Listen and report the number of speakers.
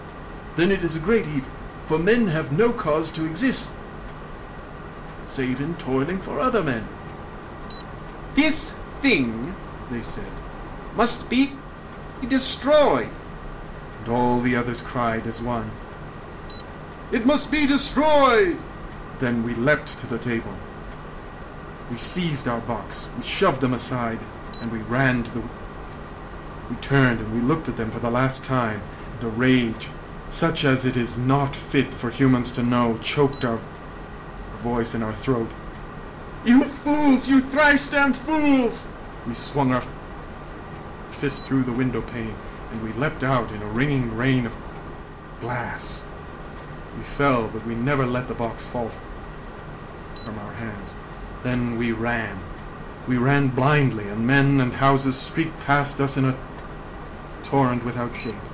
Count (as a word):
one